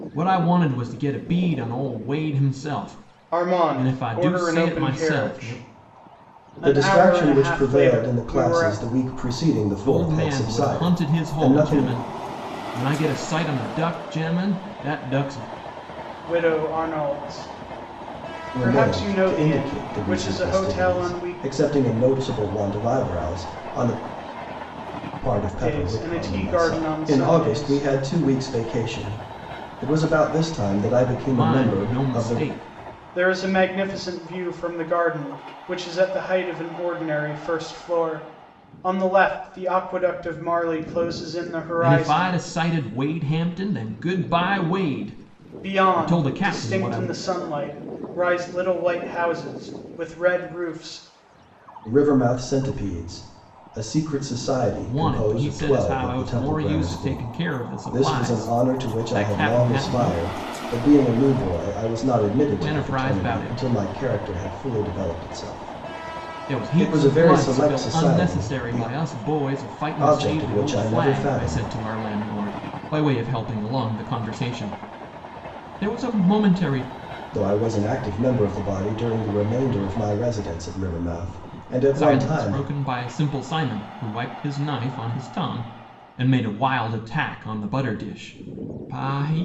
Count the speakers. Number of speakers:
3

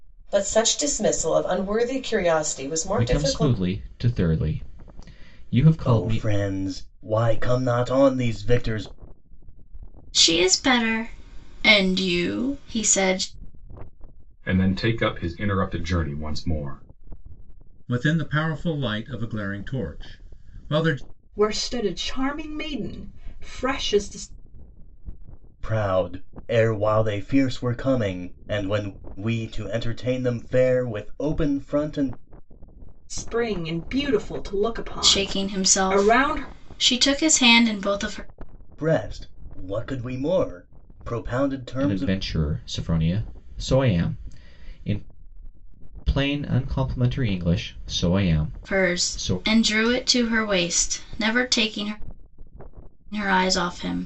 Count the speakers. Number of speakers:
7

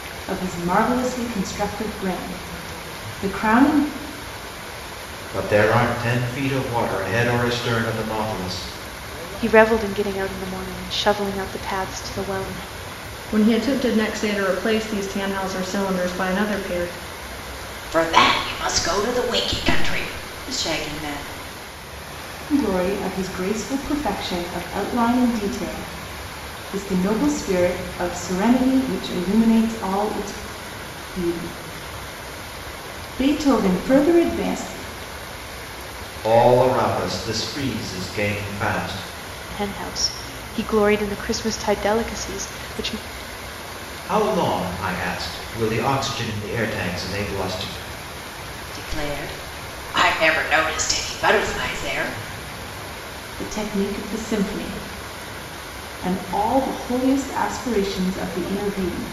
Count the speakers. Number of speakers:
5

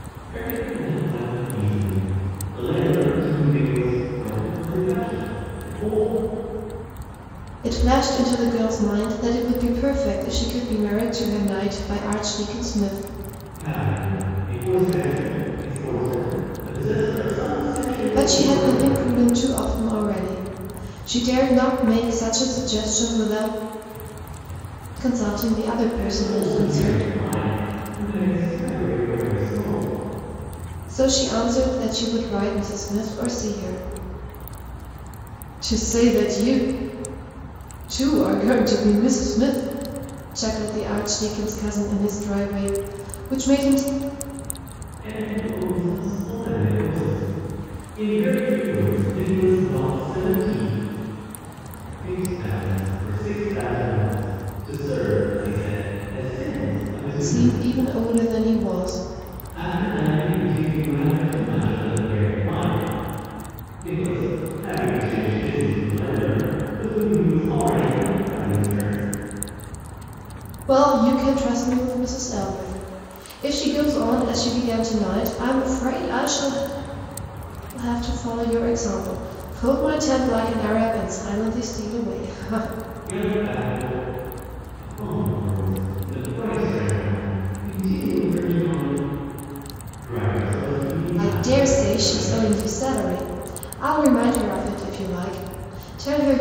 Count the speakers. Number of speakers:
2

